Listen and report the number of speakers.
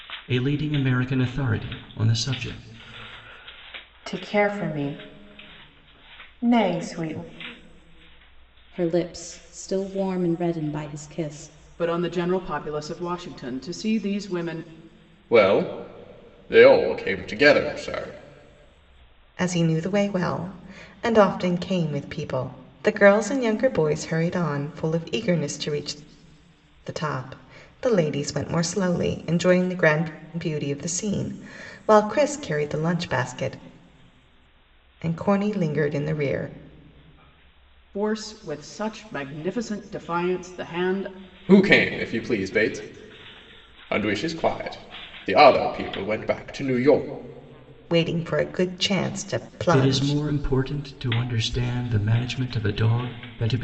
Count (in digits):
6